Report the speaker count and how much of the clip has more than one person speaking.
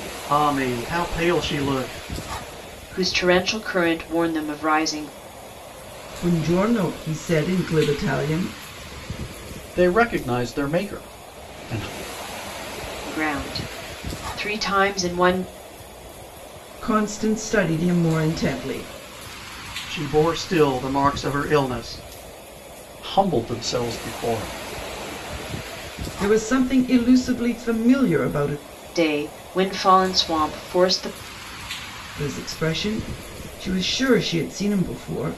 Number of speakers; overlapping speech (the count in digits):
4, no overlap